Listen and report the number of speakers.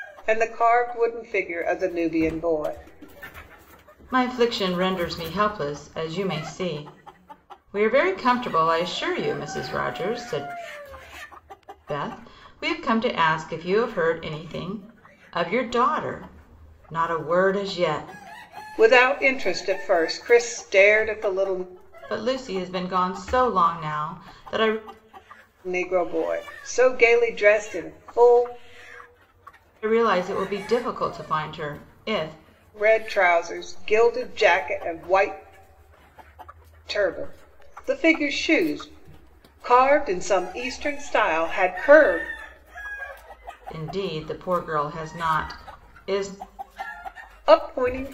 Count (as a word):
two